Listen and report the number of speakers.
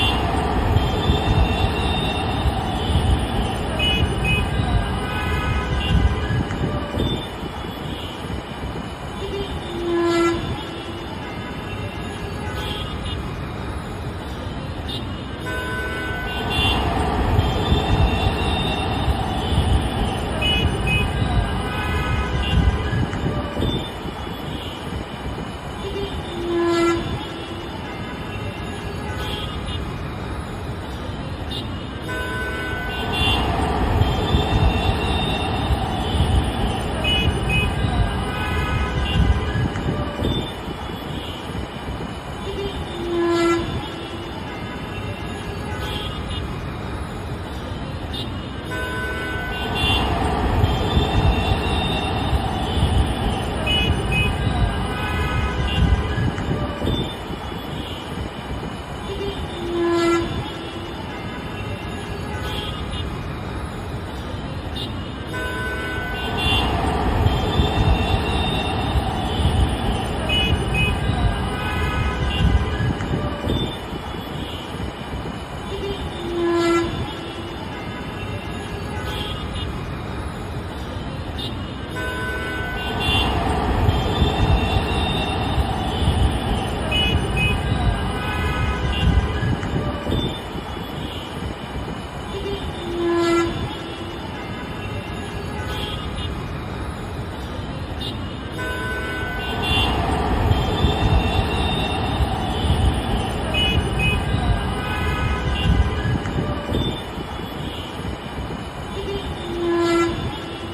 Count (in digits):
0